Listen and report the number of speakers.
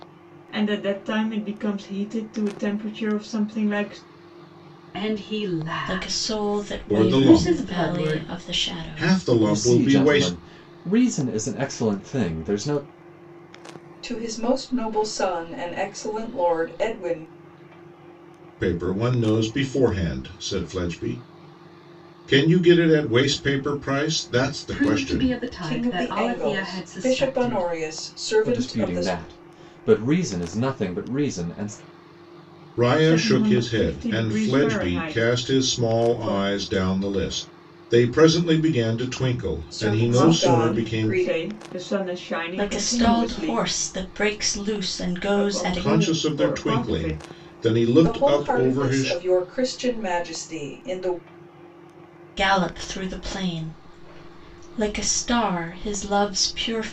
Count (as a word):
six